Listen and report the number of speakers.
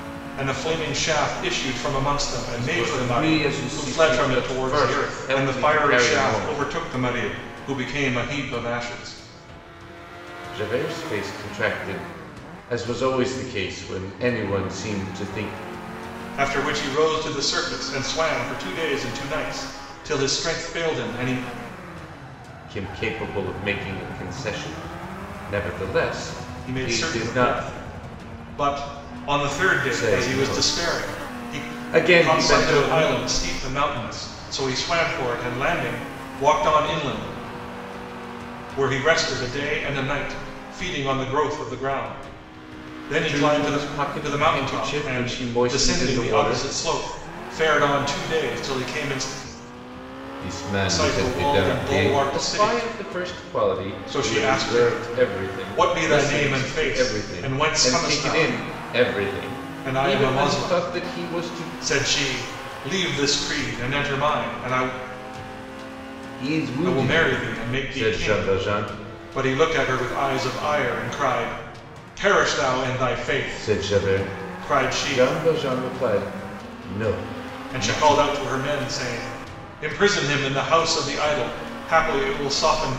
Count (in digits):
2